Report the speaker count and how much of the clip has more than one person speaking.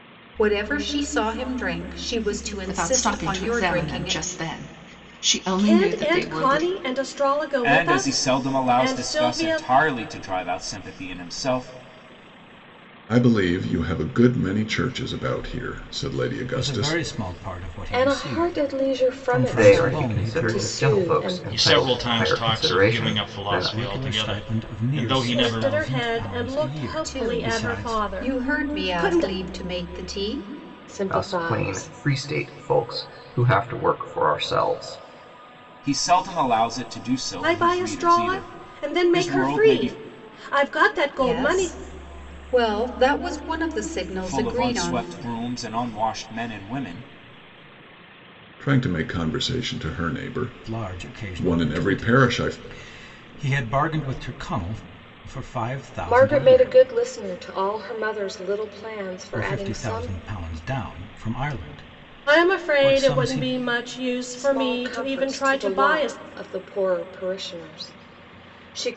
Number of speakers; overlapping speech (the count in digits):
9, about 41%